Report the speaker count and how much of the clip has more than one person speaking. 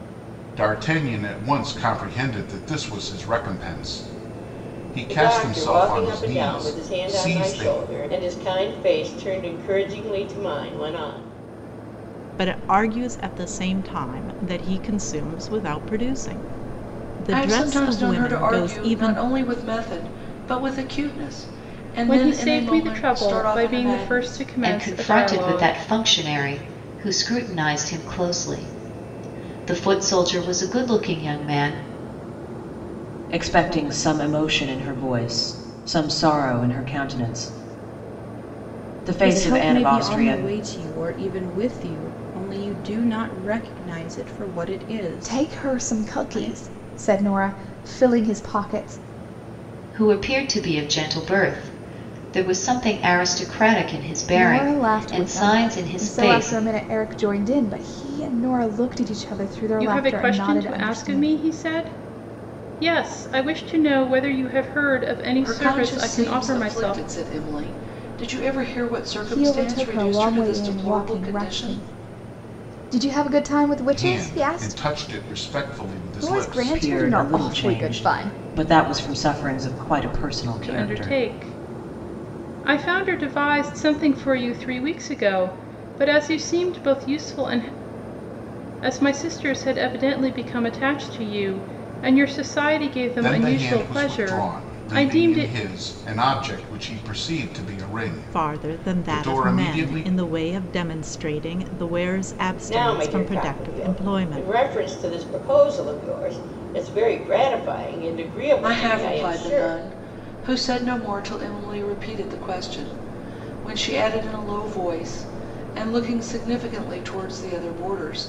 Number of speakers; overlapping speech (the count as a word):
nine, about 26%